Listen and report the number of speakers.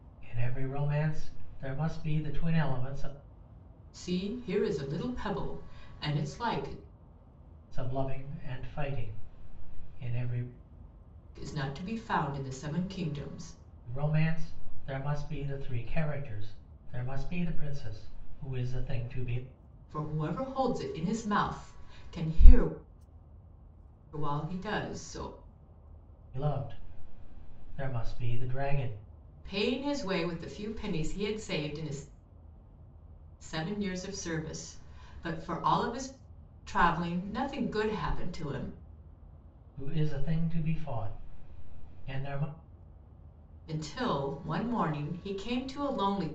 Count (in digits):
2